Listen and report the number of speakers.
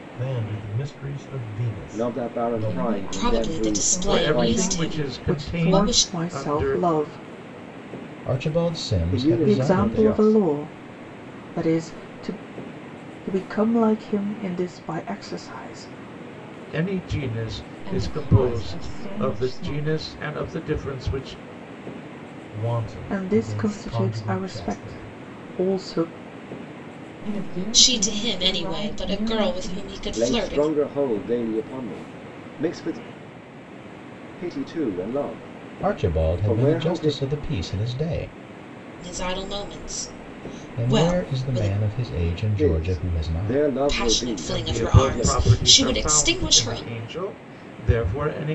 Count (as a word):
seven